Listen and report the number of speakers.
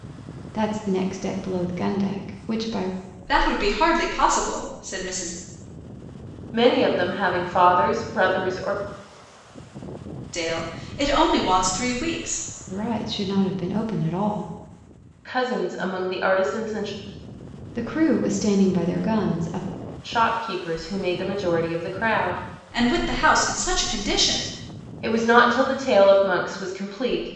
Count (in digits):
3